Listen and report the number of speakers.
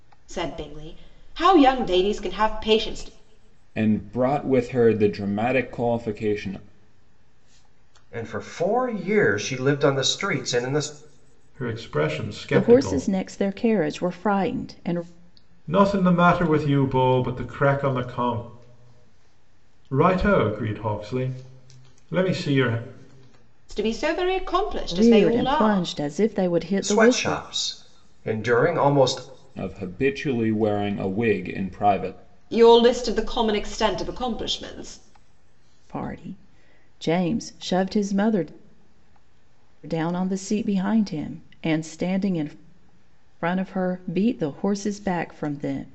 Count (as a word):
five